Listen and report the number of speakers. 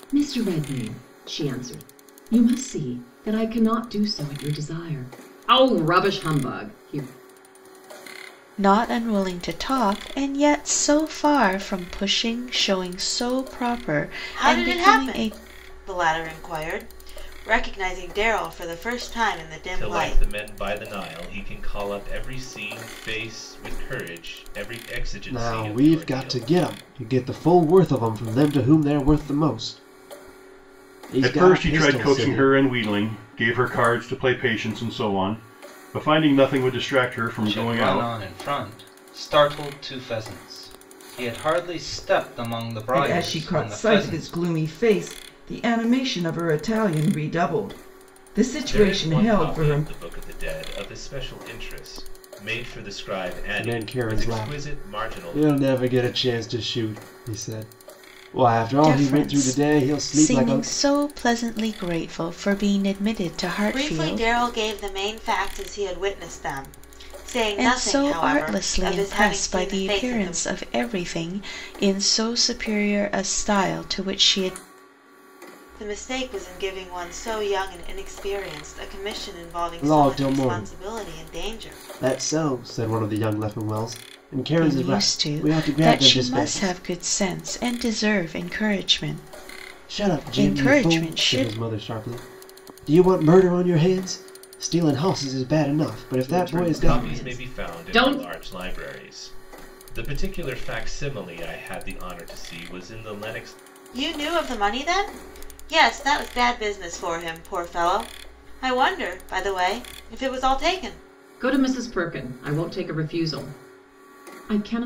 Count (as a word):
eight